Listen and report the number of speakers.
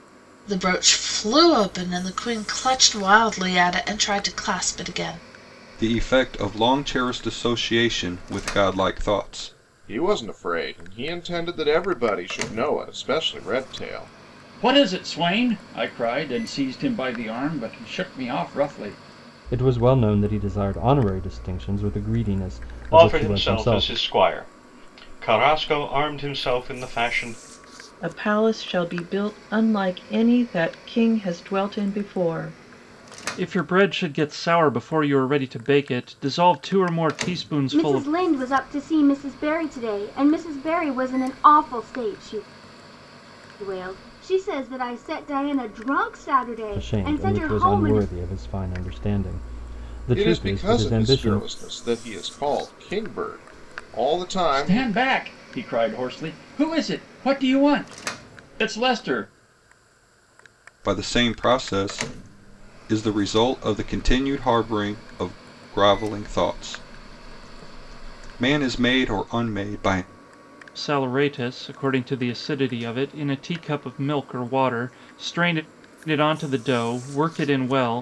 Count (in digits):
9